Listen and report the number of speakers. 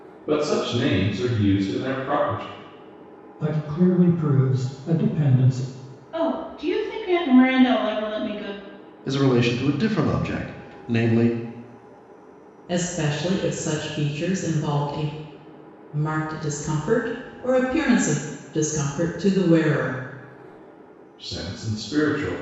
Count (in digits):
5